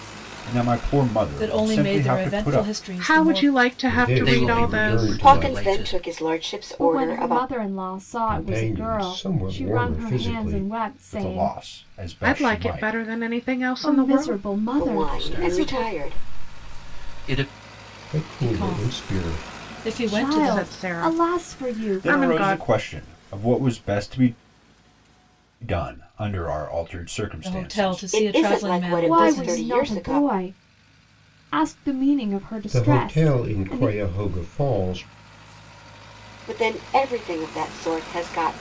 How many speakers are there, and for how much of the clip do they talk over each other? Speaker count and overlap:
7, about 48%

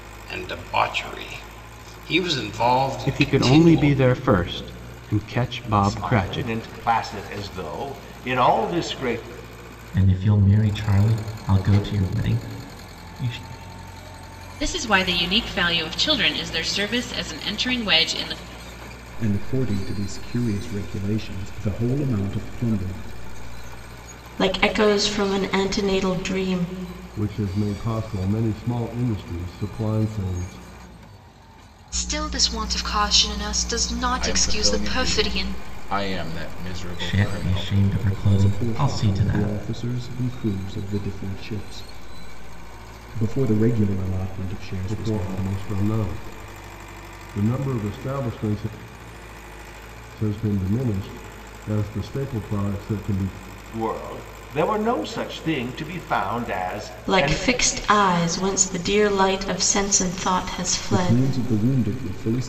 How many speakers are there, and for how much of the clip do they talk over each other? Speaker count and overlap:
10, about 11%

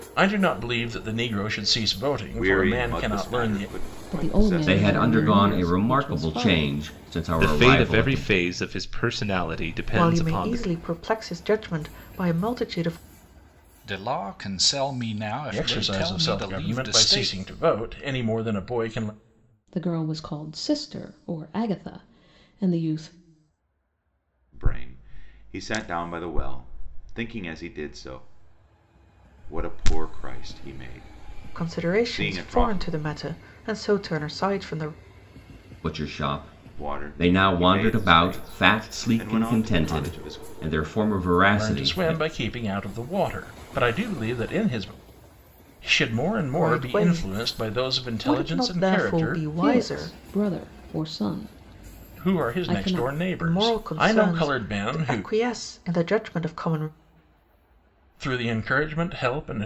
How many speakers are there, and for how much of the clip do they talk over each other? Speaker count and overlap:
7, about 34%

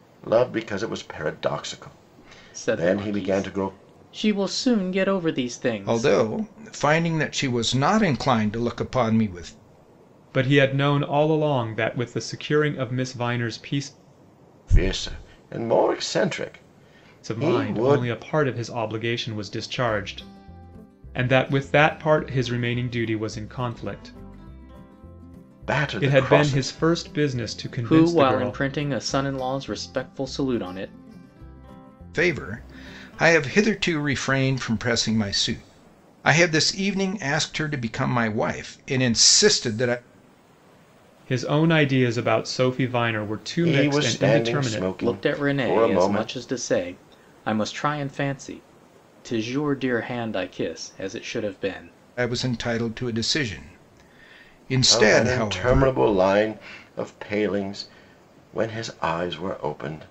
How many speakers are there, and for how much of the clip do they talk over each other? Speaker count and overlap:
4, about 13%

